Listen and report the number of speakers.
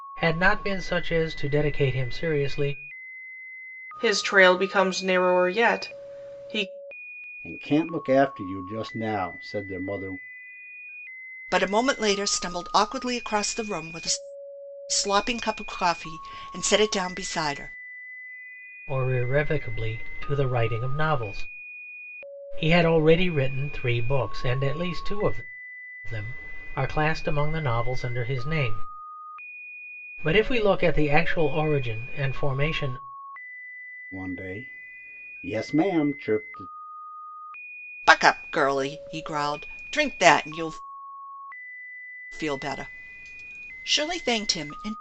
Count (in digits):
4